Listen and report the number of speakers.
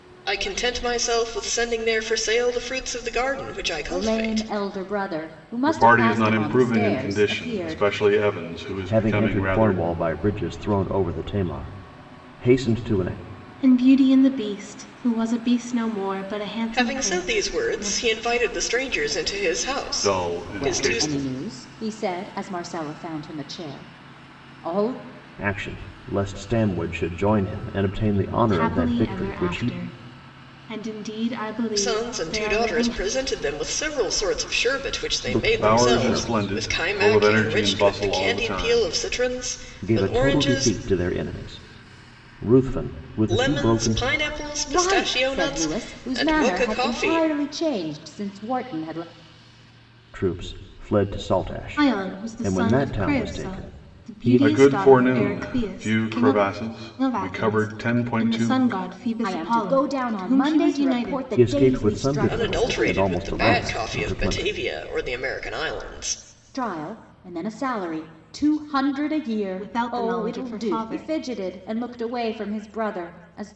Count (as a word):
five